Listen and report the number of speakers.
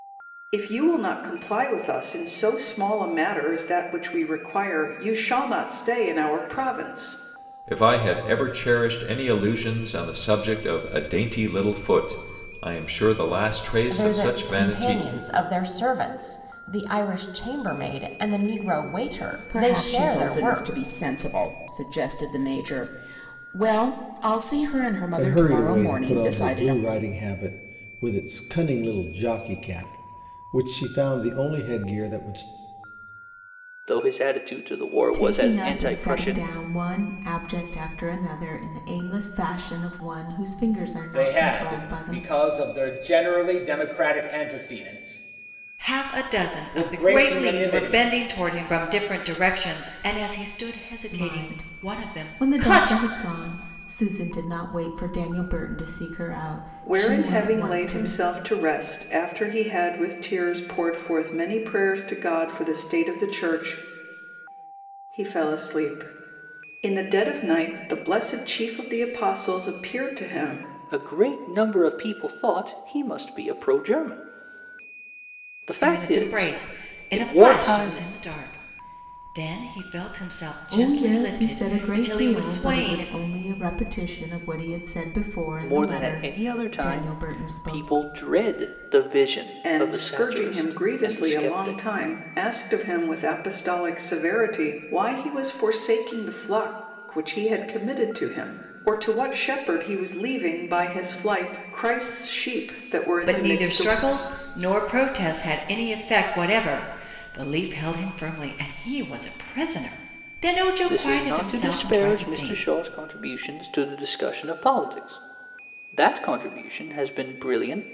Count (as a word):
nine